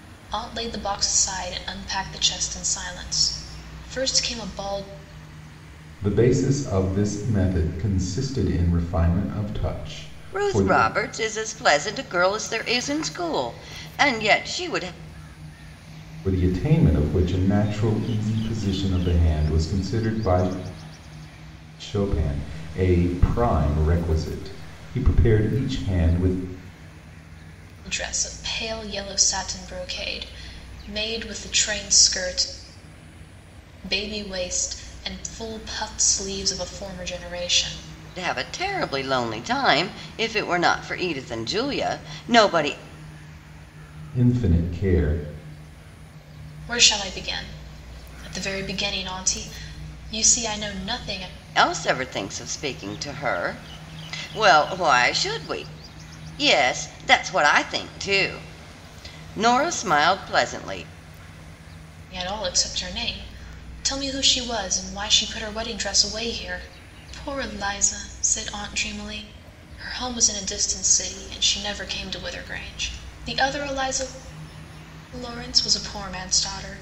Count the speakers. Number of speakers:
3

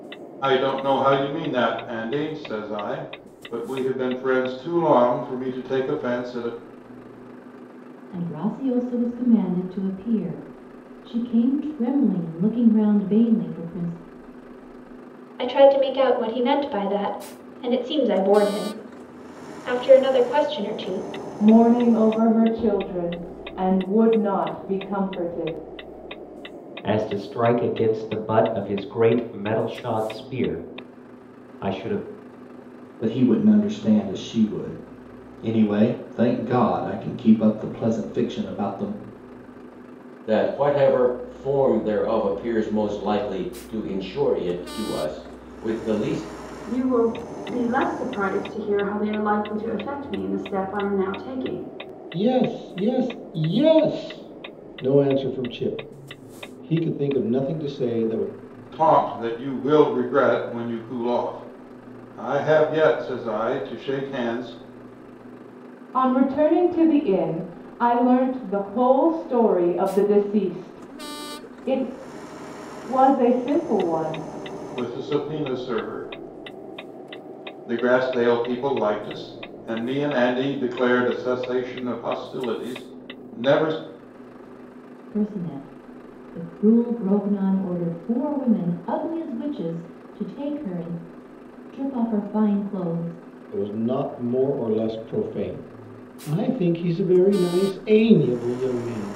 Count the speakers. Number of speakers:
9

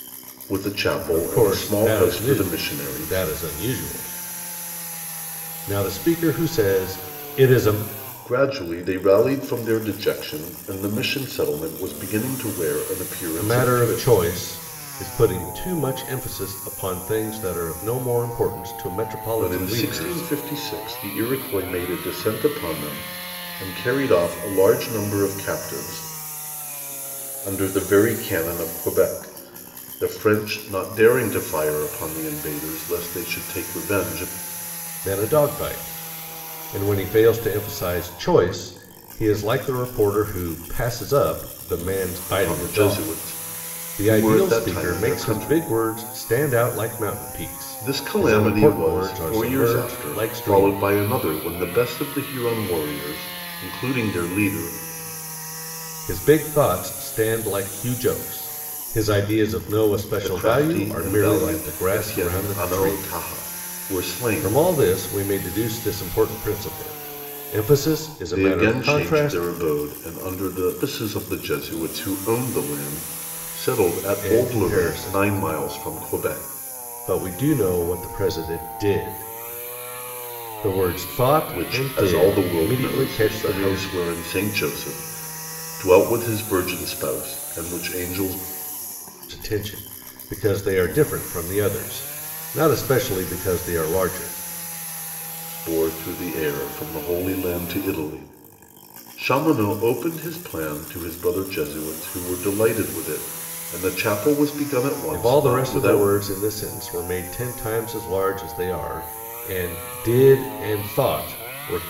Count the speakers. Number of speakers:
2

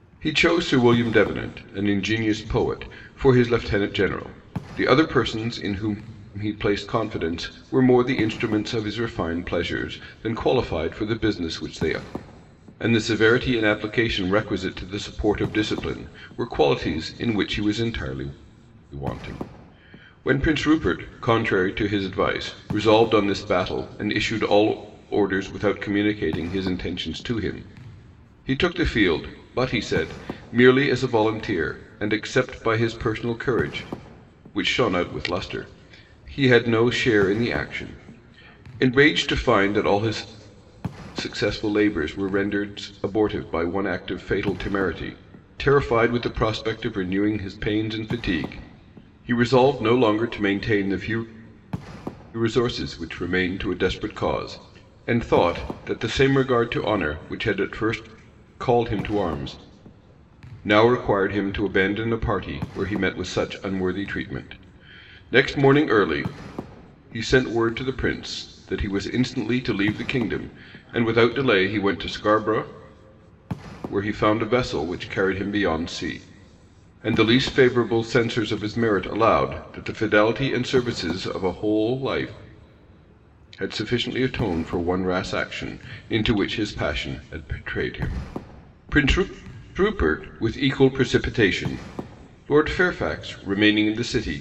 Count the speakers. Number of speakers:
1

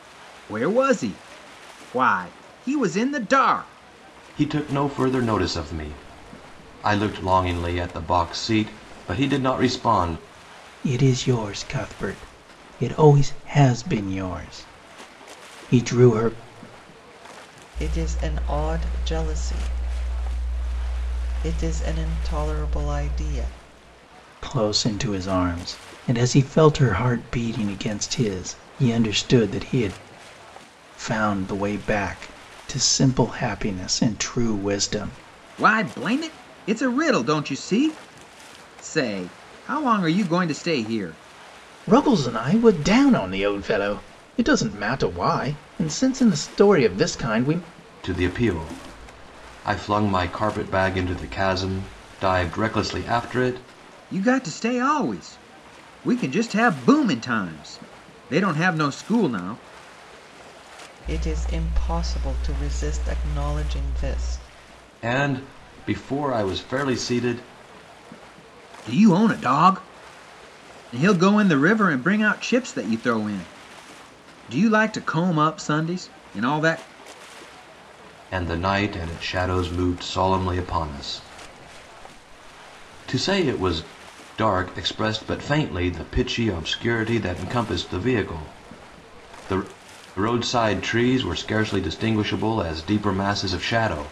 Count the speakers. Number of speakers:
4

